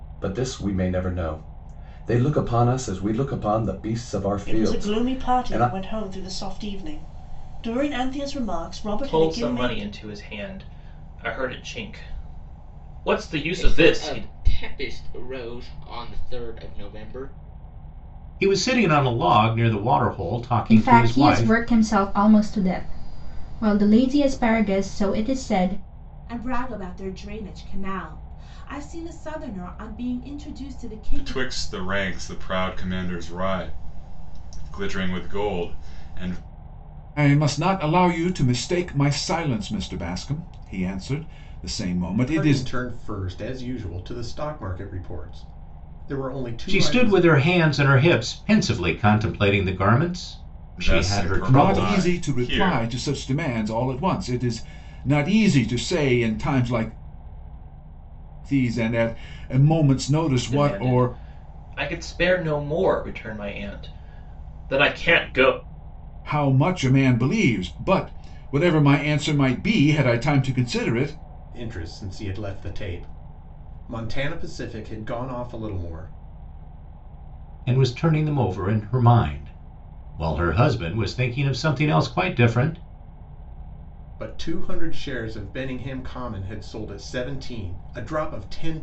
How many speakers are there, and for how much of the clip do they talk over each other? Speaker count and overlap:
10, about 9%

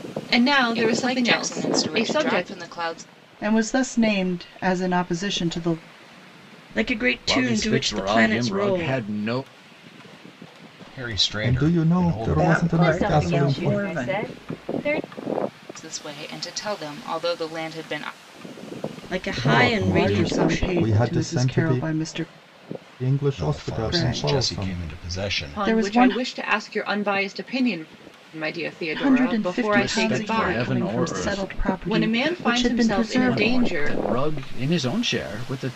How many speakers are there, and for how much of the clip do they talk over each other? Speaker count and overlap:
9, about 46%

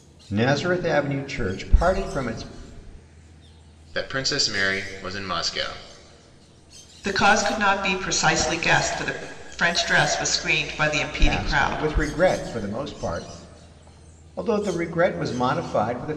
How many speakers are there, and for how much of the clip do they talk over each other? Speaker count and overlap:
3, about 5%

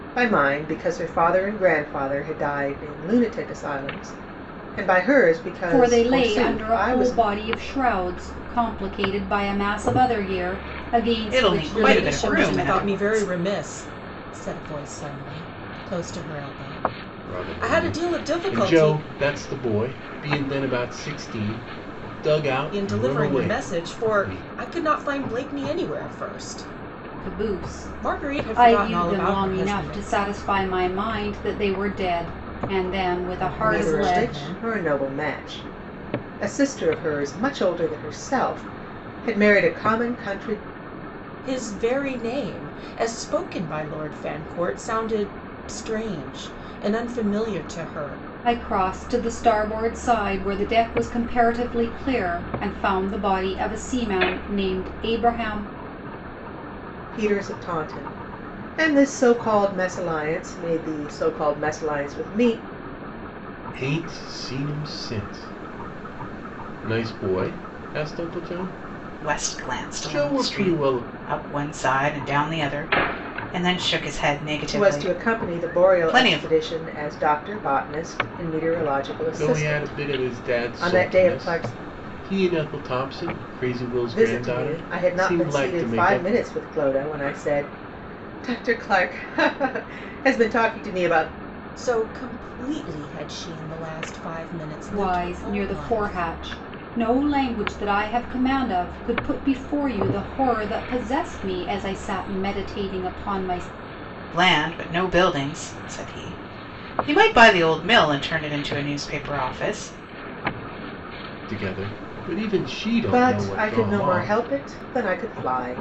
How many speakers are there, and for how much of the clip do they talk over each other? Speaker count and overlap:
5, about 19%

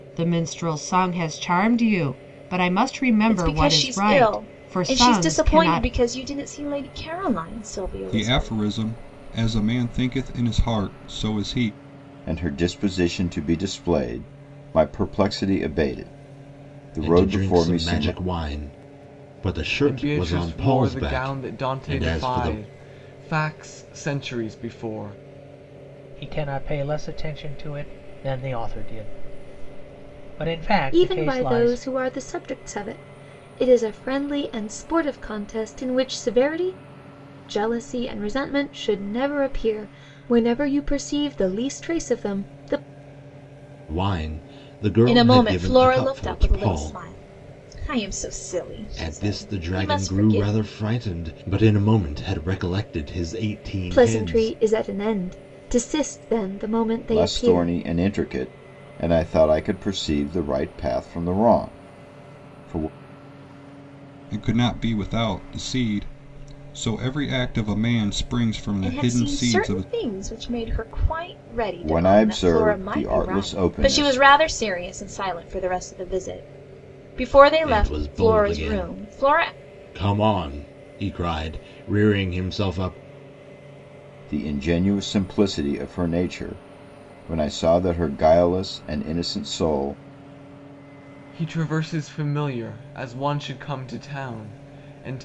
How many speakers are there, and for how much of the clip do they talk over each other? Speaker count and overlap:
8, about 20%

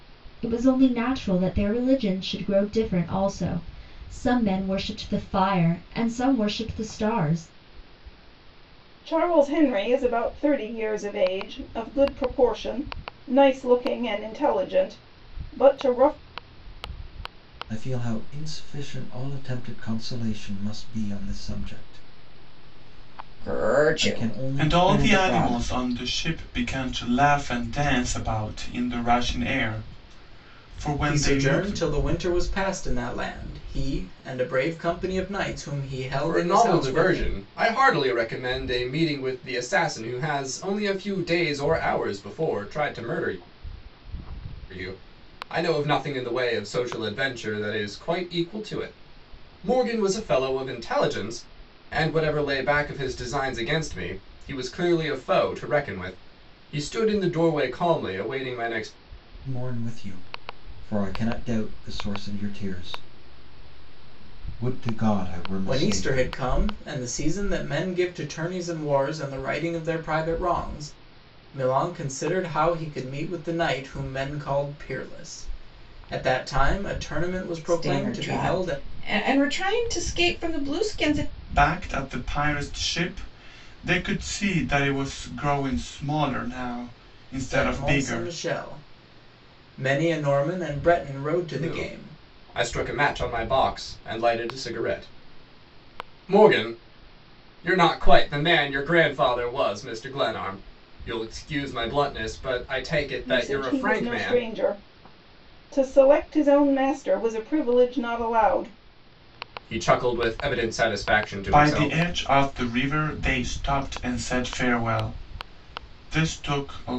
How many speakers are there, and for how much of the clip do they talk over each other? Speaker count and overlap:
7, about 8%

